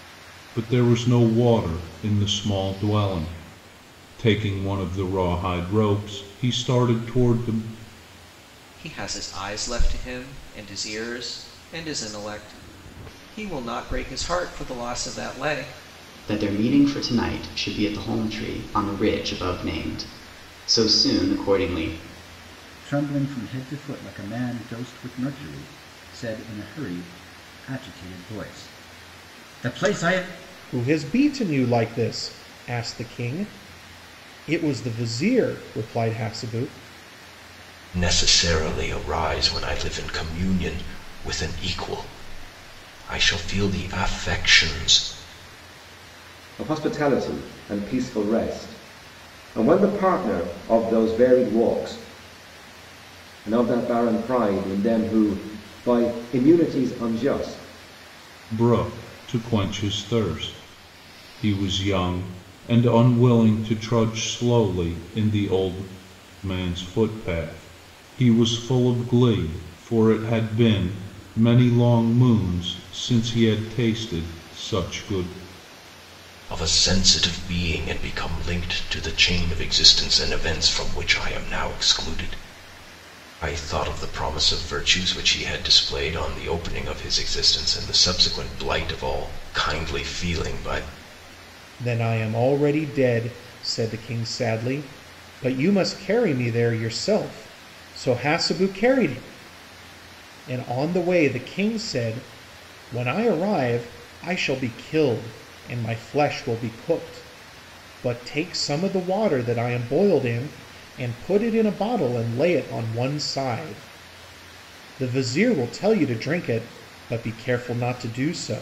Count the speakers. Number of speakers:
7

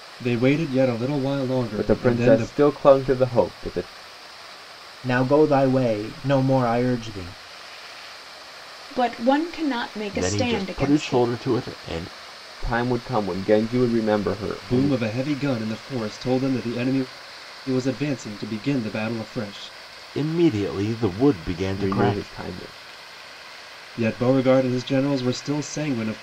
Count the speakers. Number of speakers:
5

